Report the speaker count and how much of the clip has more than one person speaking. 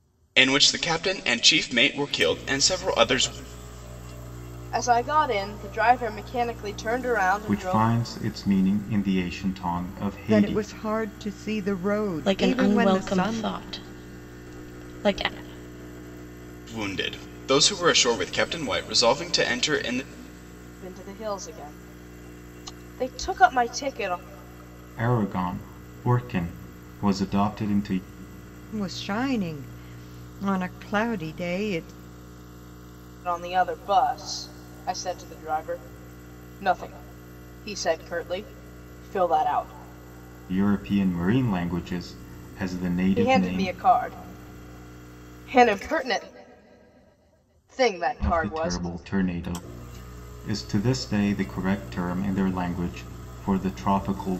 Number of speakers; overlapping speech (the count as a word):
five, about 7%